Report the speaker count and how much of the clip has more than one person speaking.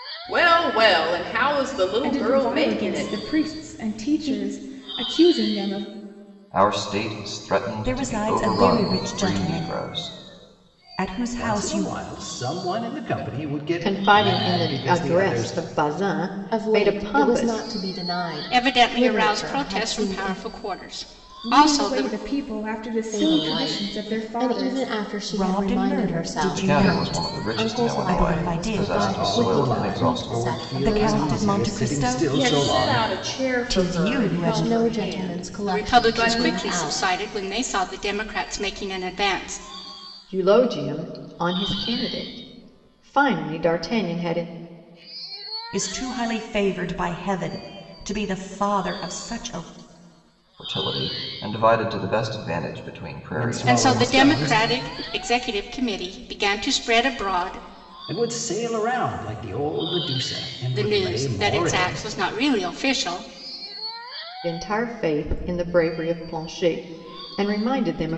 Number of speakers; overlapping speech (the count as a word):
eight, about 40%